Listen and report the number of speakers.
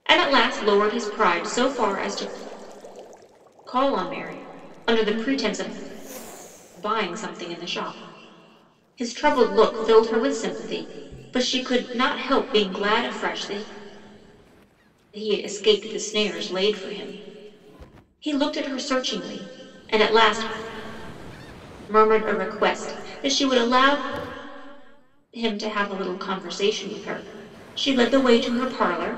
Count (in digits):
1